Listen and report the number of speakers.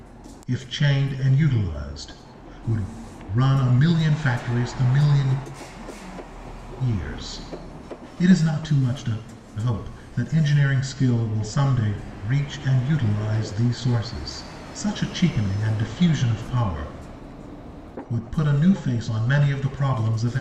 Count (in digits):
1